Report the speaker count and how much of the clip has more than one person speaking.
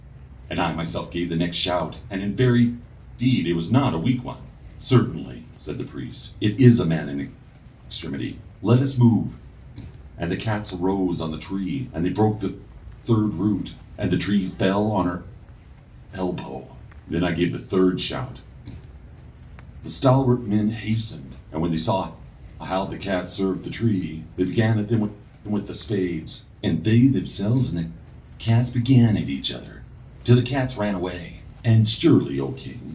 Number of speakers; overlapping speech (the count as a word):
one, no overlap